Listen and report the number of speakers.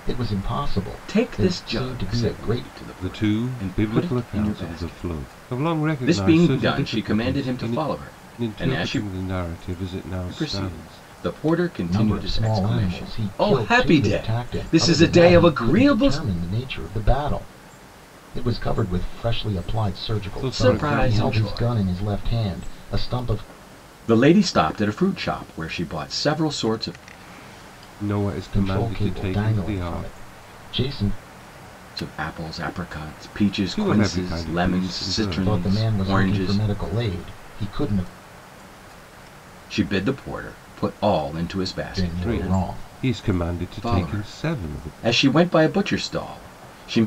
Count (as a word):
three